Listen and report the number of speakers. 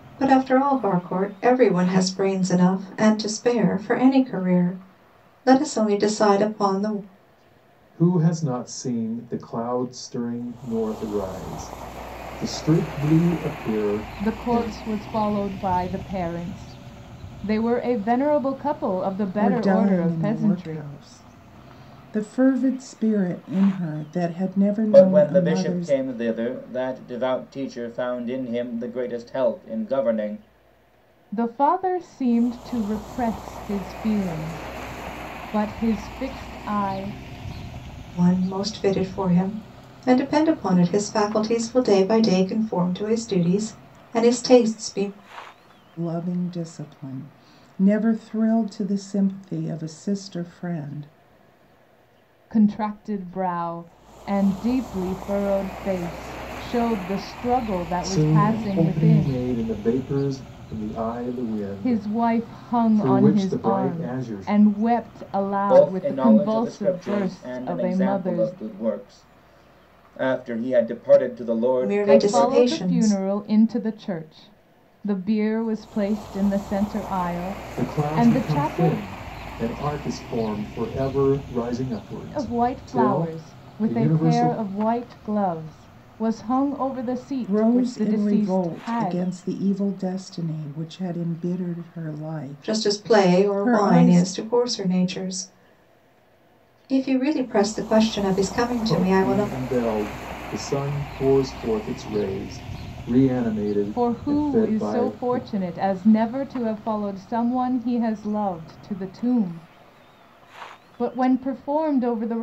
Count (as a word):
five